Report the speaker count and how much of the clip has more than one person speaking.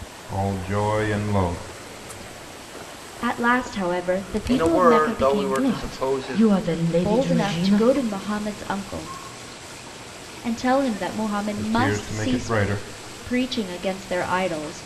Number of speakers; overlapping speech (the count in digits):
4, about 27%